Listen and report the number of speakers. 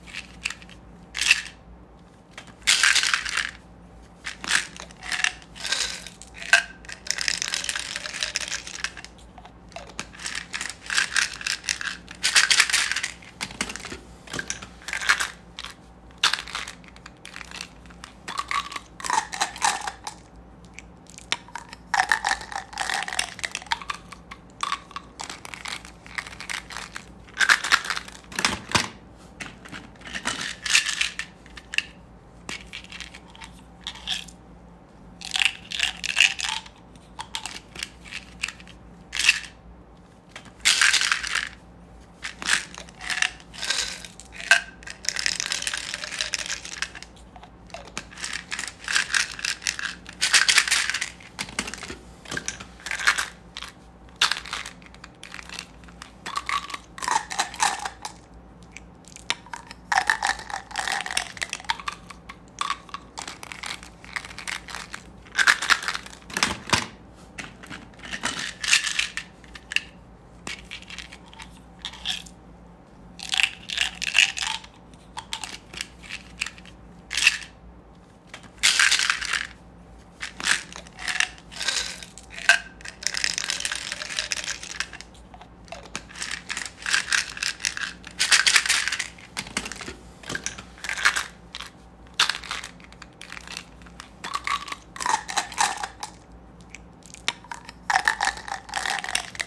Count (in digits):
0